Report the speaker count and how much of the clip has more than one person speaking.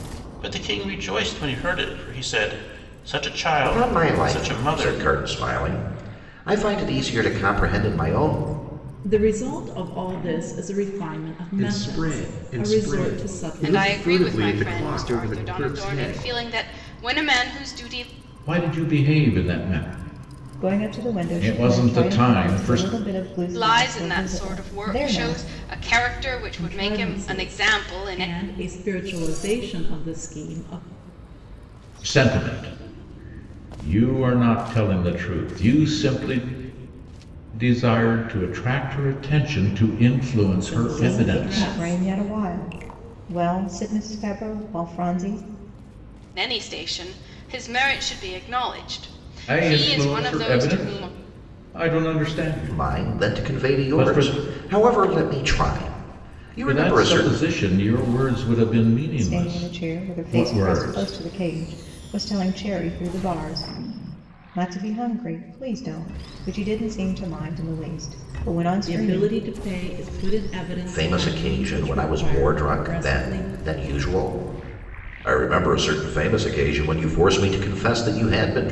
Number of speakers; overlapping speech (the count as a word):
seven, about 29%